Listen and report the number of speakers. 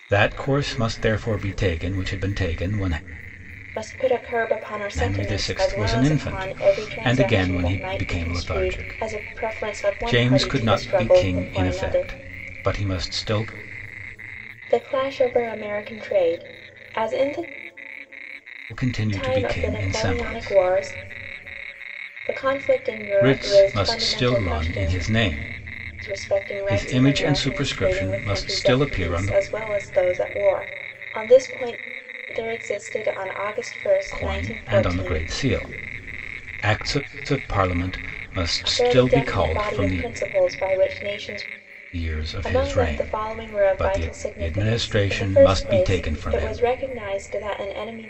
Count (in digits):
2